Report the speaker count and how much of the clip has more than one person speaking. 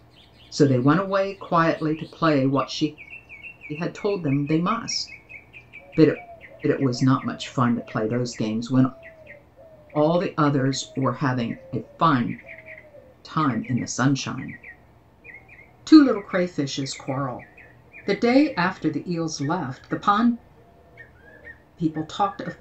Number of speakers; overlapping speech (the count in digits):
1, no overlap